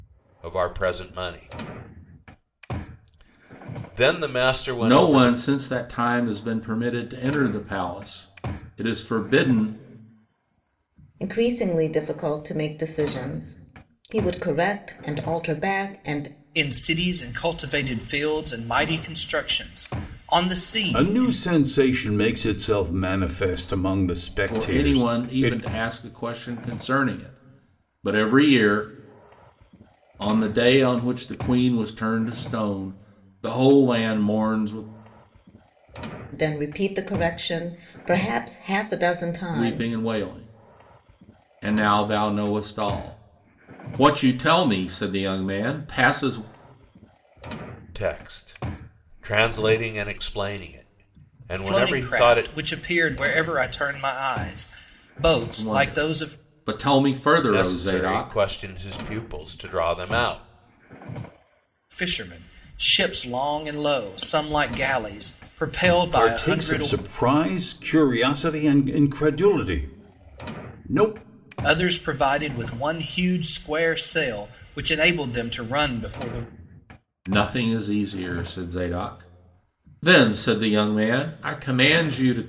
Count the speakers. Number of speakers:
five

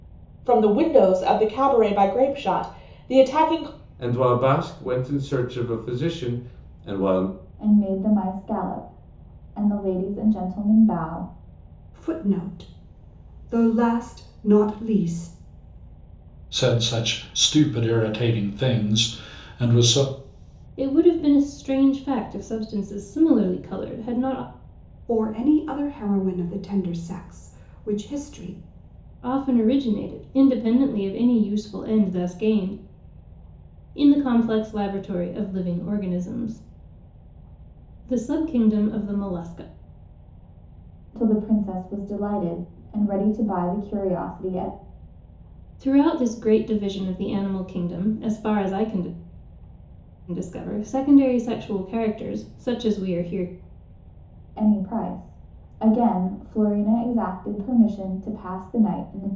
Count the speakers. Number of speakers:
six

